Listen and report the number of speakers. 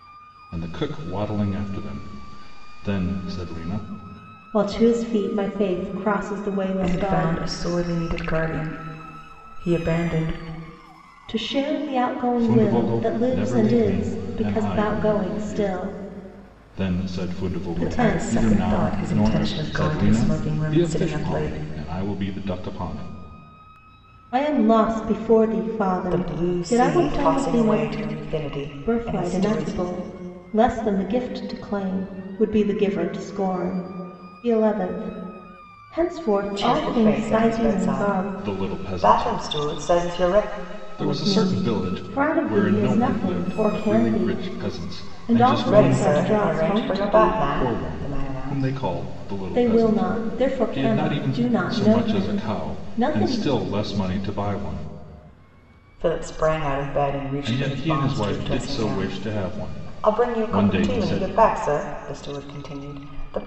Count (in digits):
3